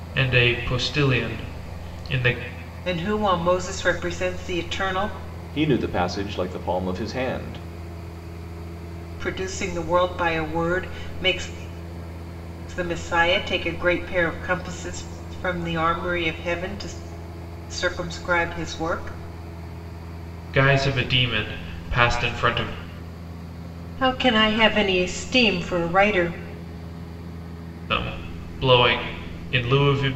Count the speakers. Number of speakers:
three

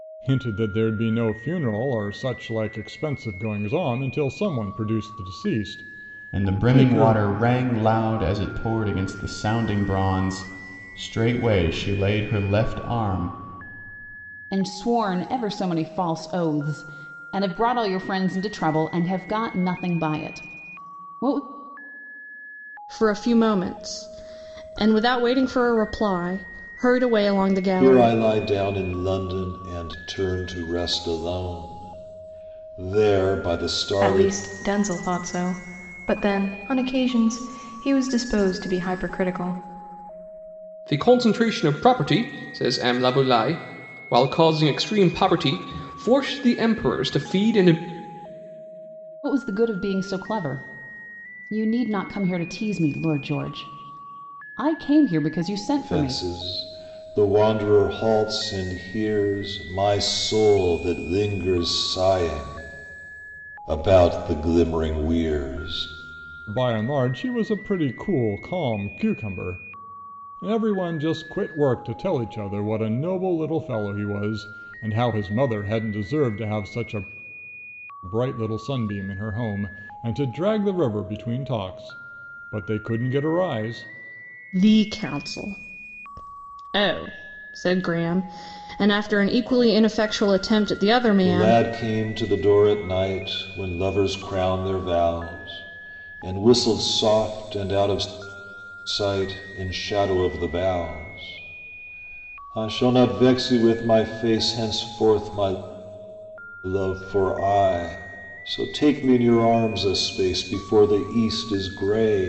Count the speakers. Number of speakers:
seven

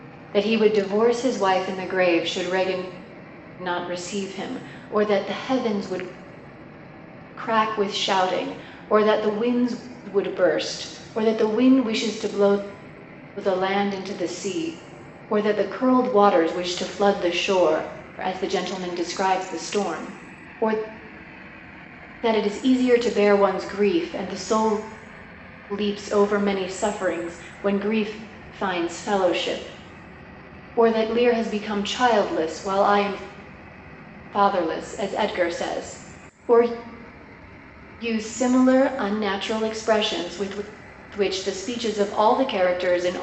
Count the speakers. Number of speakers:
one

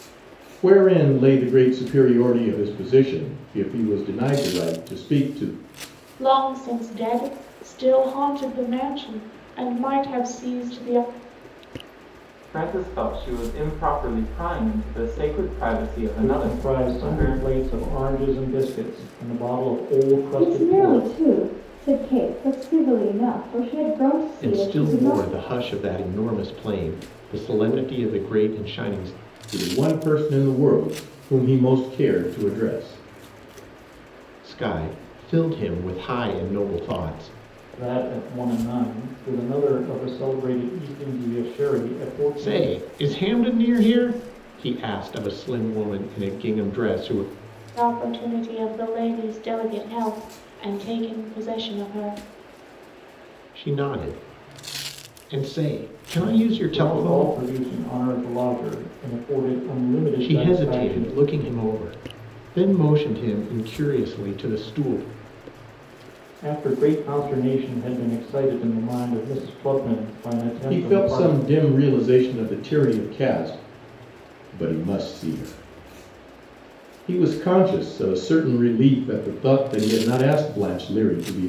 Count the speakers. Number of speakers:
six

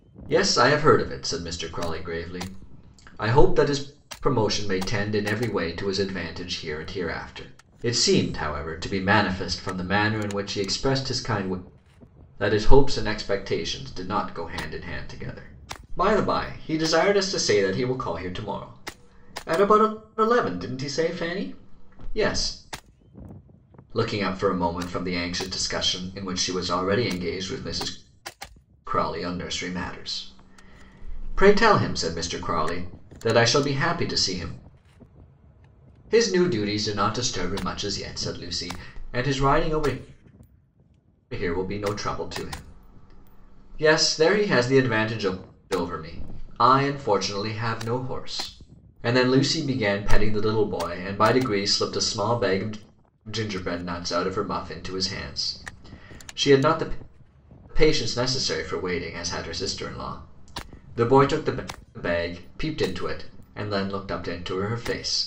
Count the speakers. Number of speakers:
one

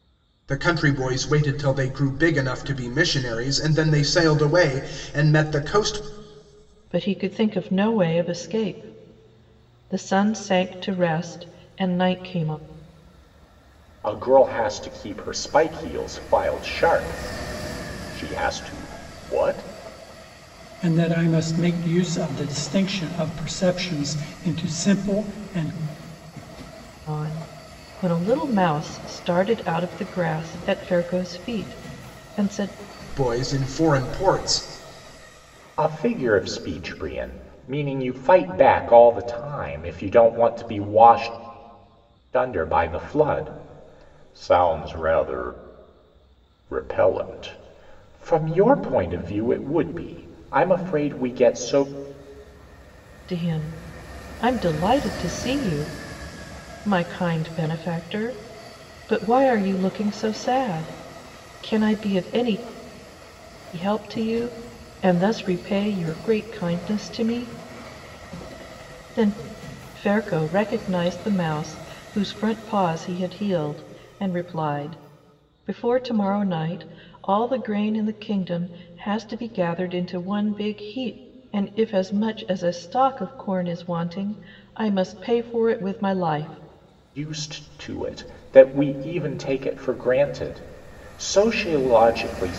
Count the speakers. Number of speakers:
four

